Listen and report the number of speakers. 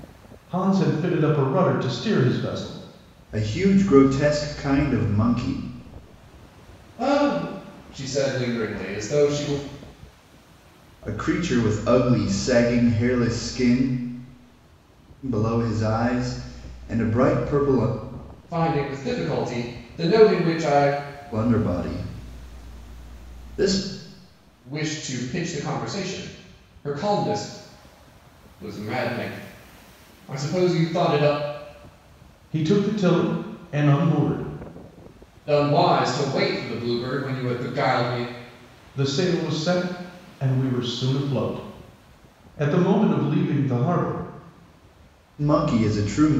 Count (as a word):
three